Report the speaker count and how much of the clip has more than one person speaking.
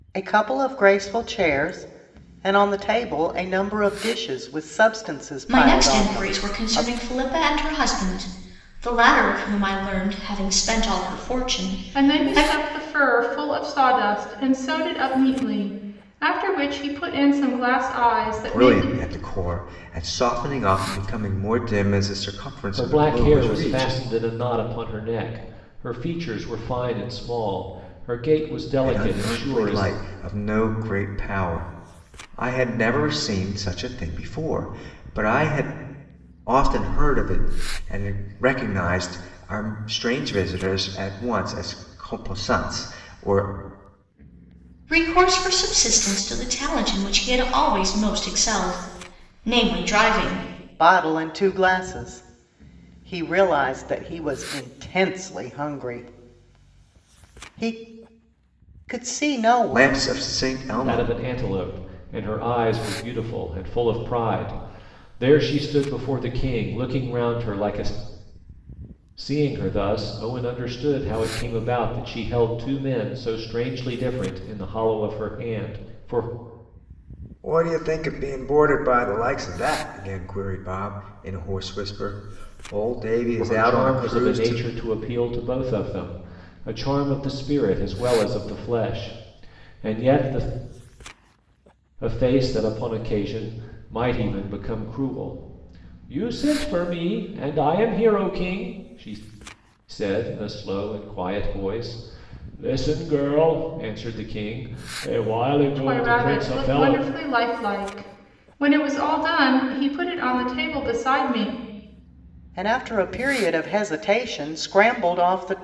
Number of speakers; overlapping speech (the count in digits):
5, about 7%